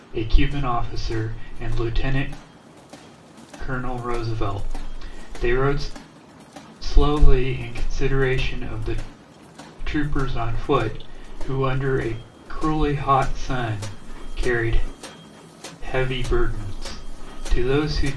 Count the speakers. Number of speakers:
1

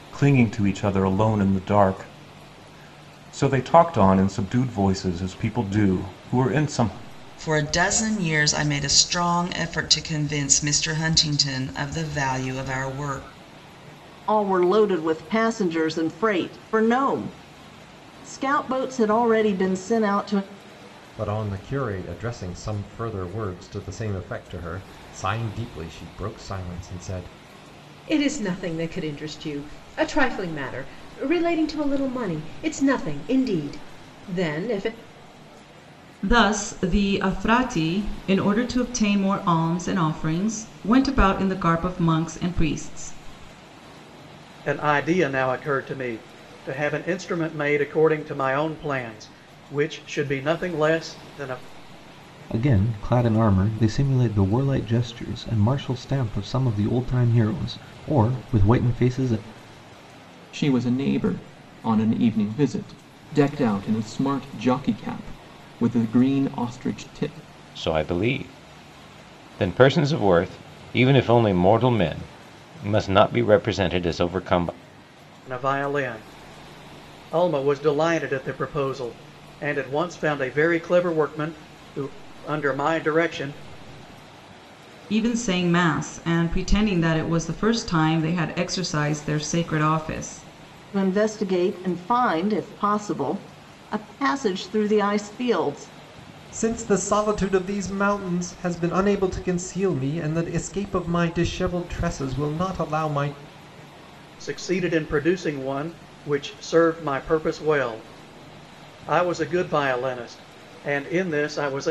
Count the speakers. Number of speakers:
10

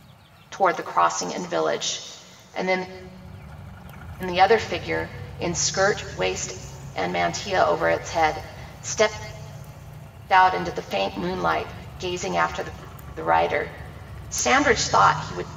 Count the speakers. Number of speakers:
1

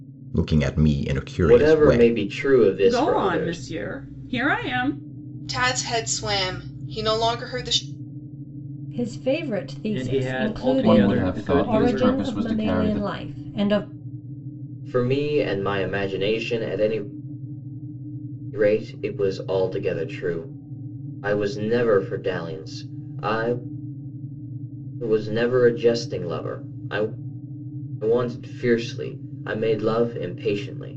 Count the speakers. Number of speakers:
7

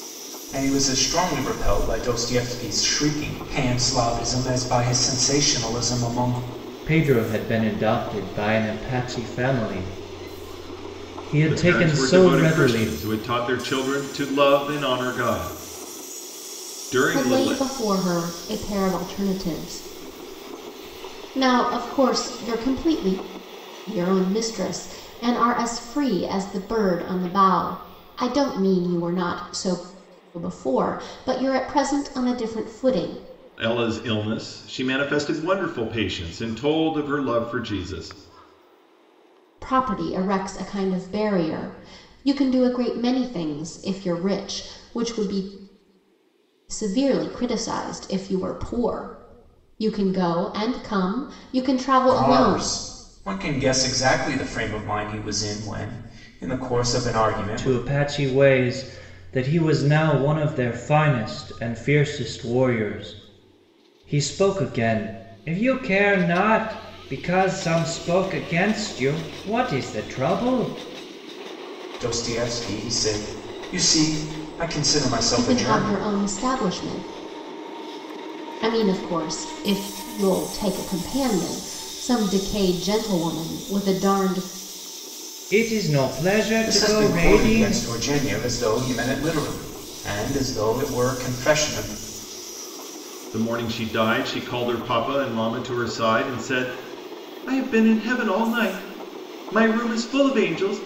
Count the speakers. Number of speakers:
4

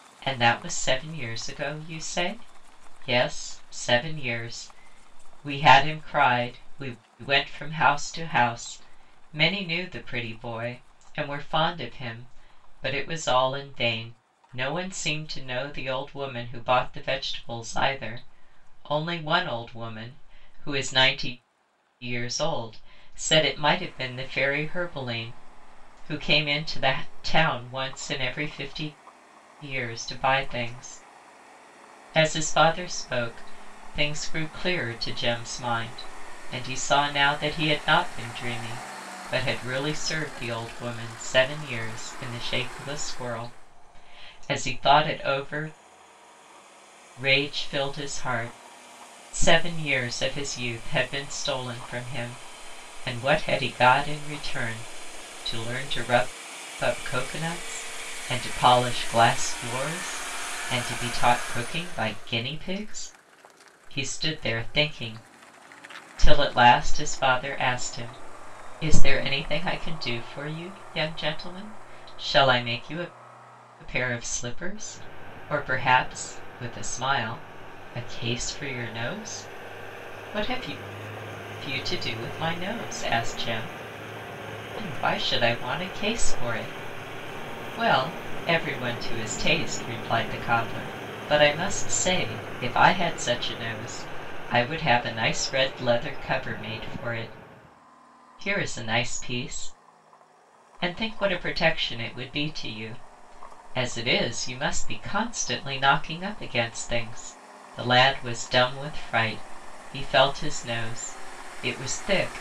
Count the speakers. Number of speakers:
1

